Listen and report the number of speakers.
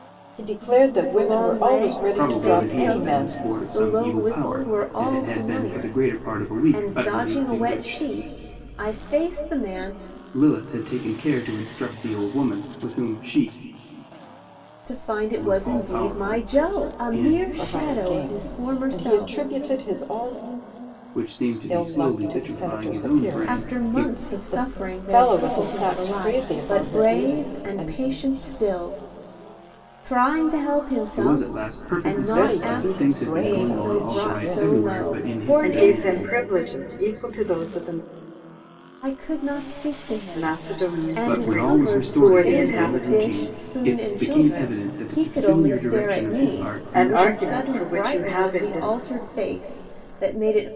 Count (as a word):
three